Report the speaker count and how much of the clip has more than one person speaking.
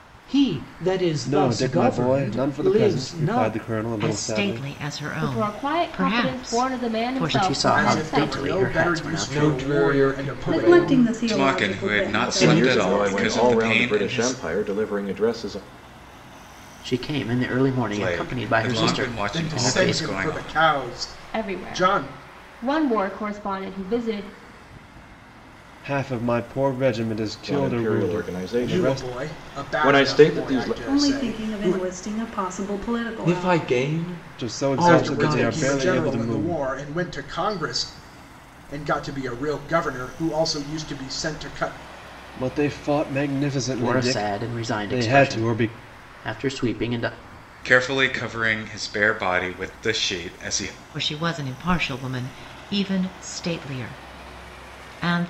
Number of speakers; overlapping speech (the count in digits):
10, about 45%